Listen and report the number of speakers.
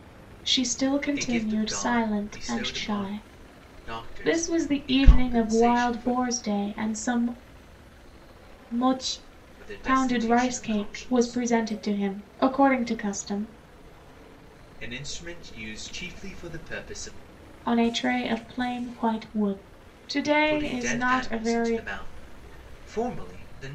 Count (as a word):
two